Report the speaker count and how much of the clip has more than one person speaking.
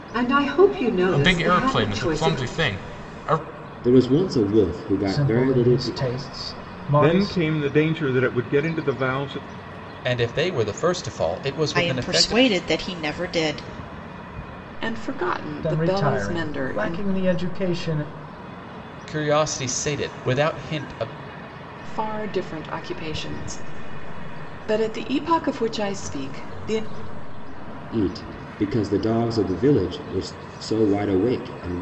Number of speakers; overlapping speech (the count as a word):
eight, about 16%